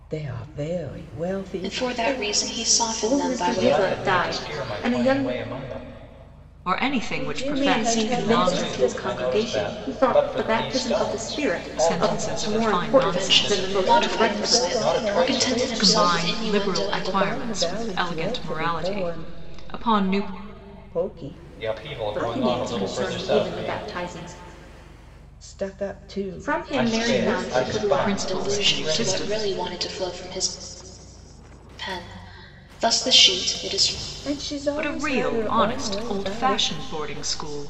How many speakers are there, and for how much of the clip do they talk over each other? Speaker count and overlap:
5, about 60%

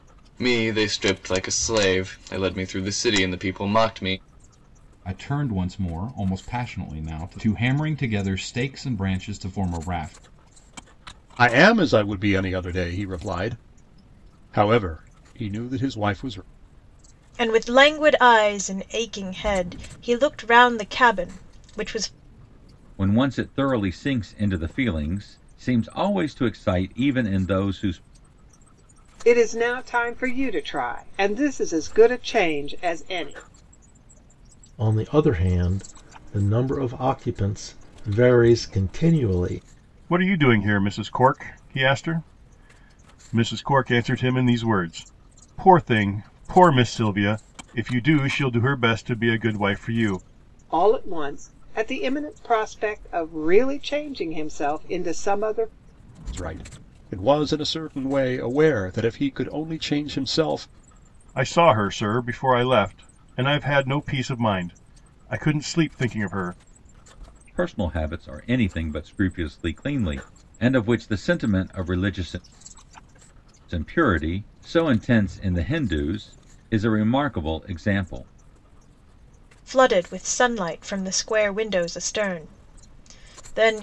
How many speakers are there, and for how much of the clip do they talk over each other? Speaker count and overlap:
8, no overlap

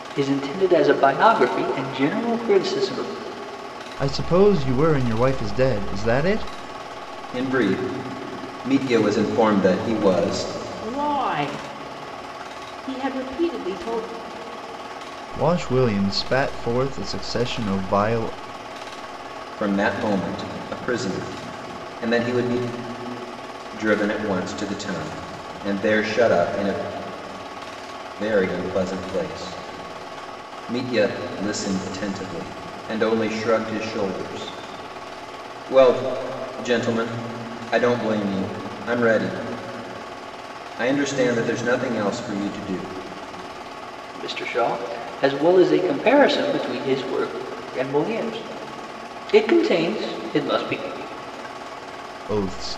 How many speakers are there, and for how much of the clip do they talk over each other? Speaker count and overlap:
4, no overlap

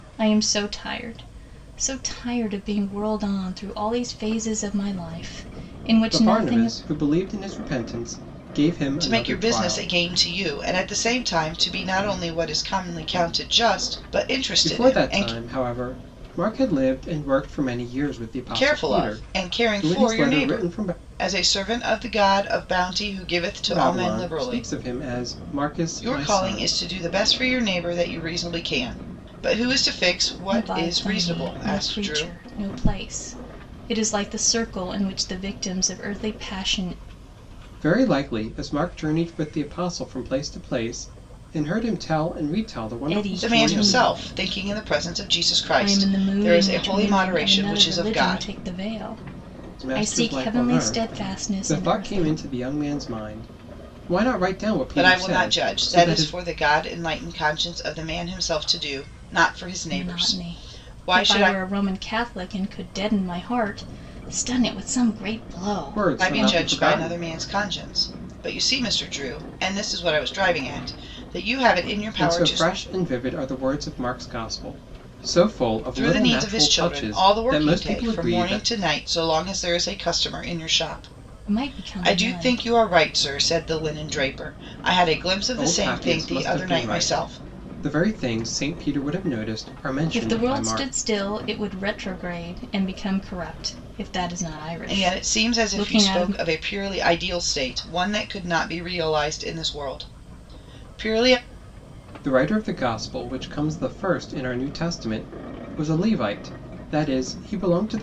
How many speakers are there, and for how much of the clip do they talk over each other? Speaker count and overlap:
3, about 26%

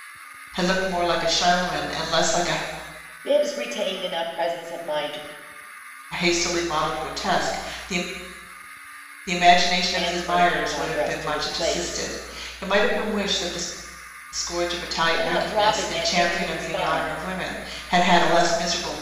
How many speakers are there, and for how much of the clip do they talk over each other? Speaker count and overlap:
2, about 22%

